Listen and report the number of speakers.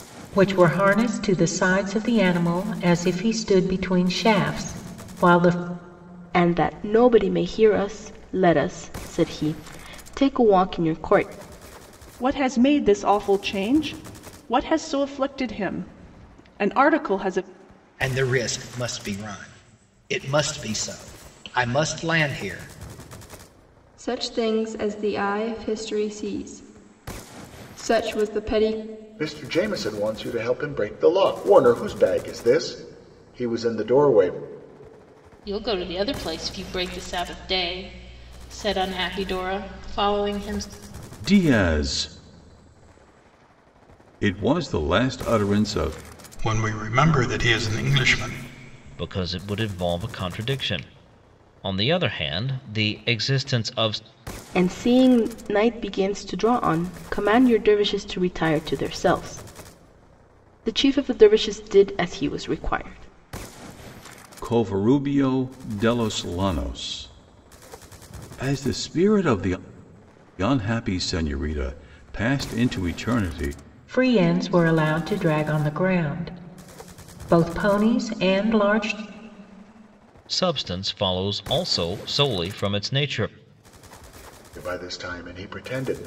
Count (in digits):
10